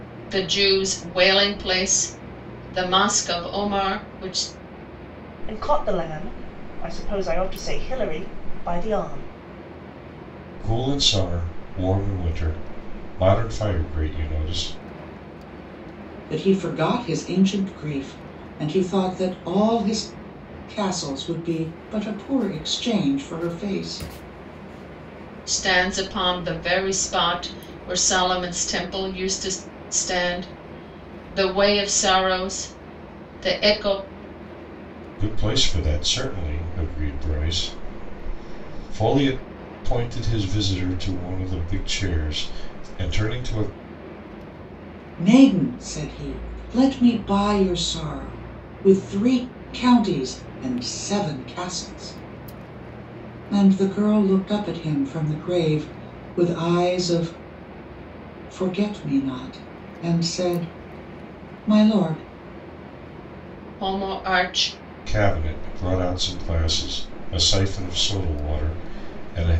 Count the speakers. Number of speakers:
4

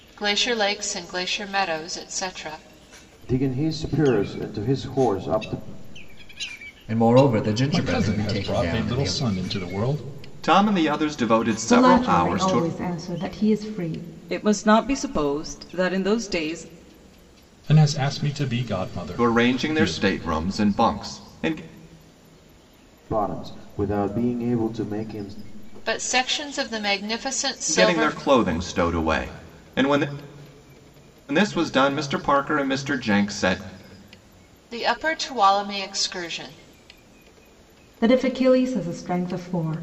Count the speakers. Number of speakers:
7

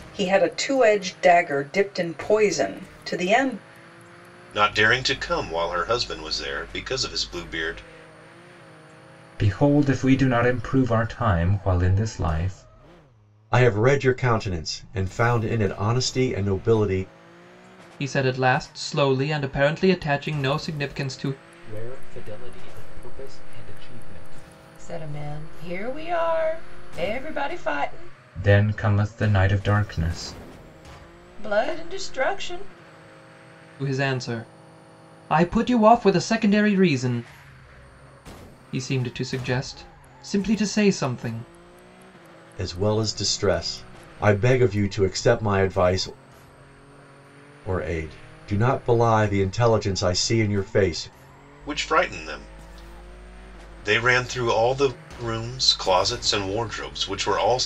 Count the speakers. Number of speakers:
7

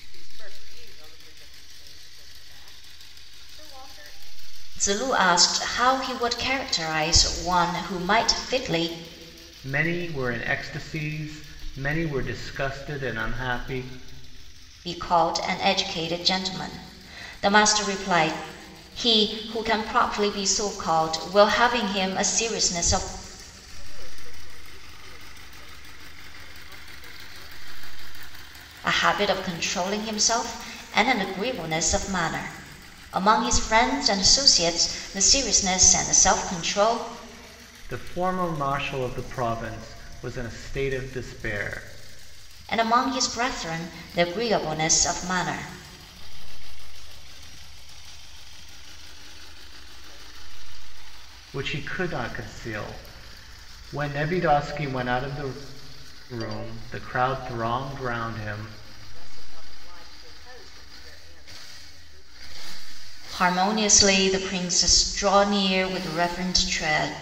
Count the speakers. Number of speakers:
3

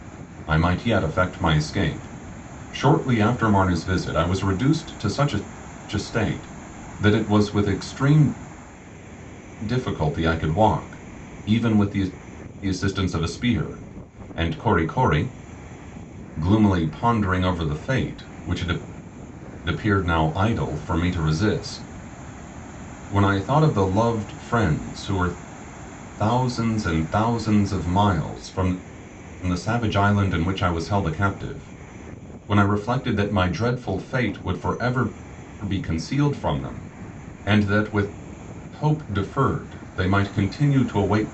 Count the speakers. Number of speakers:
1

